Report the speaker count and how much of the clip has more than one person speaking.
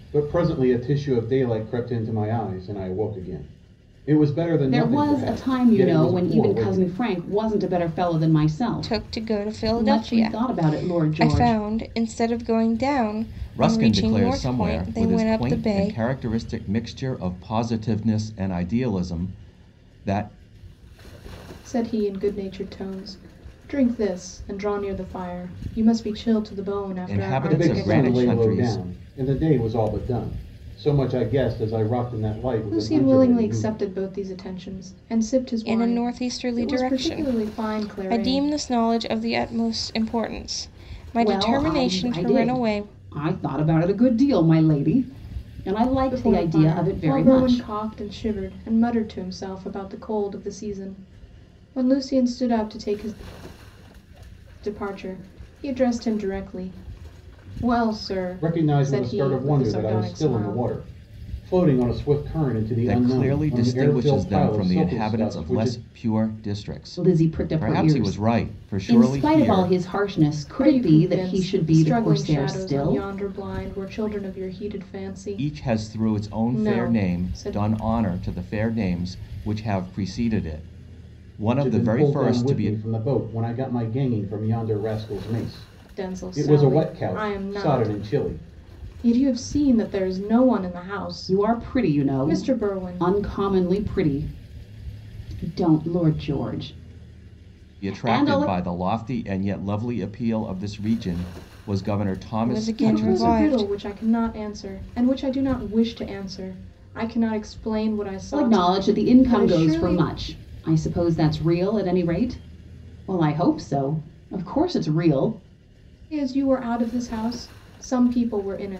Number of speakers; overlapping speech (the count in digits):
5, about 33%